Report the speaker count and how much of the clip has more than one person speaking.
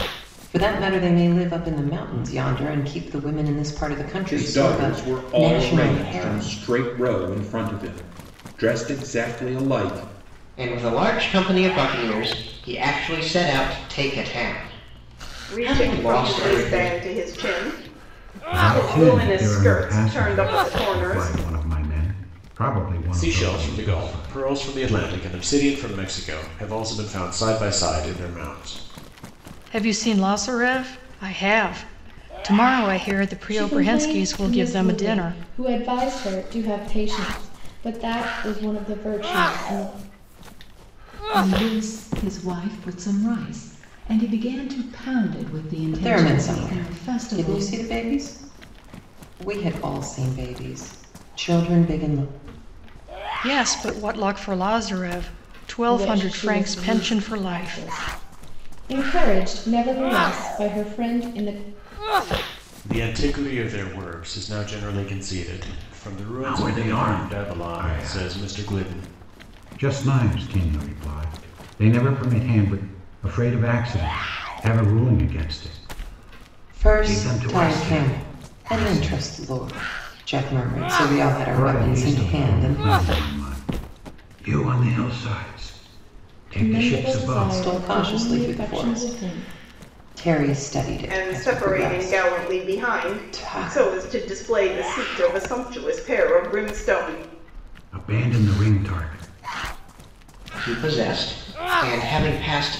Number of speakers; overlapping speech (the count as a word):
nine, about 25%